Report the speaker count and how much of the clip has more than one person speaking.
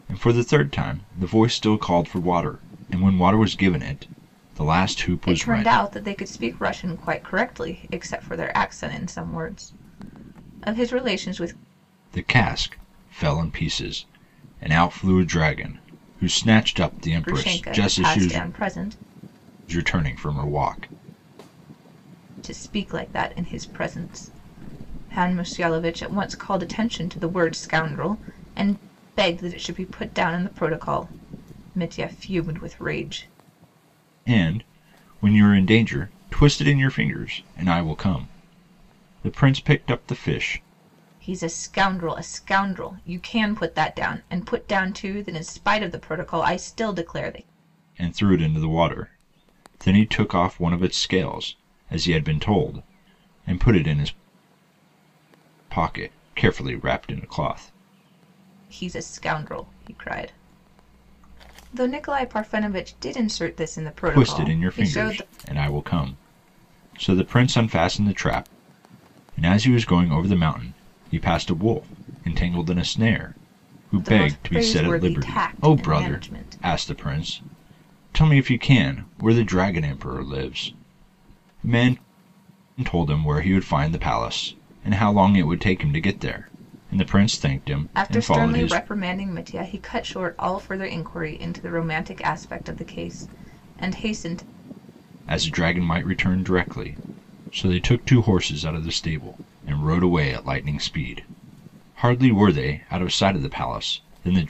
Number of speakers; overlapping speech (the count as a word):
two, about 6%